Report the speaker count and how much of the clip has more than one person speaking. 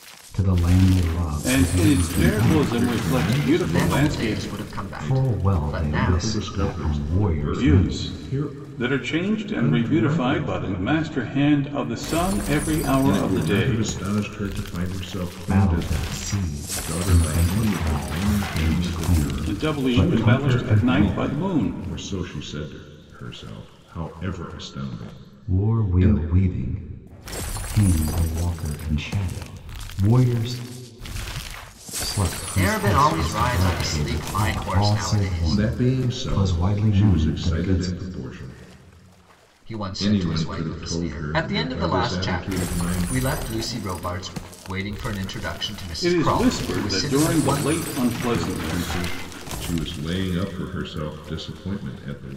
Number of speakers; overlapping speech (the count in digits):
4, about 51%